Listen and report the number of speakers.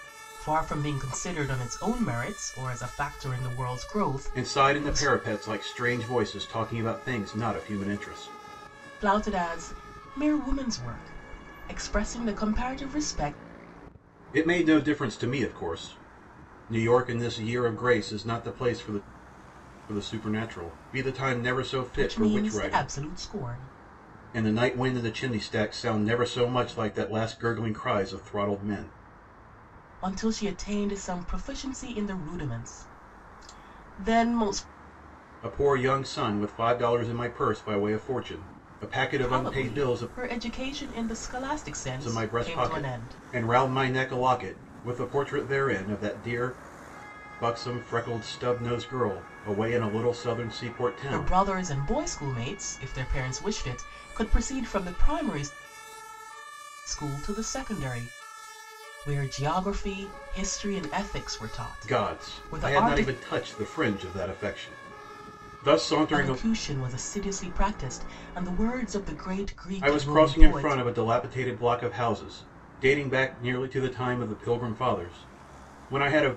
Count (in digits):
2